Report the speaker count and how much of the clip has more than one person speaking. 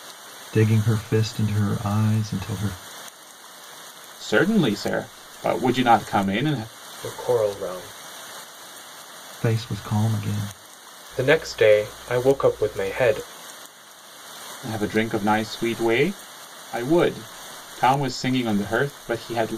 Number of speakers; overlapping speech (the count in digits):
3, no overlap